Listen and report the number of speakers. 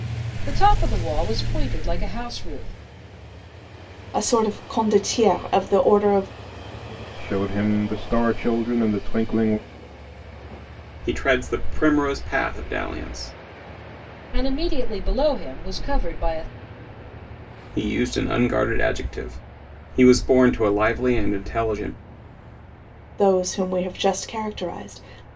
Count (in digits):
4